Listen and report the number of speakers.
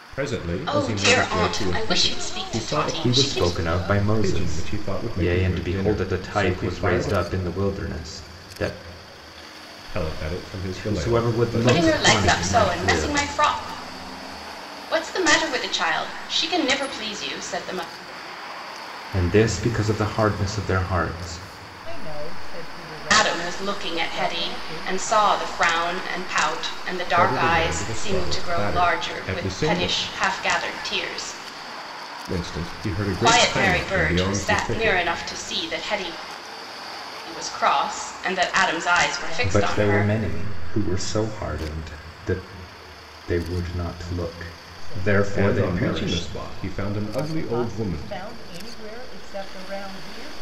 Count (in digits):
4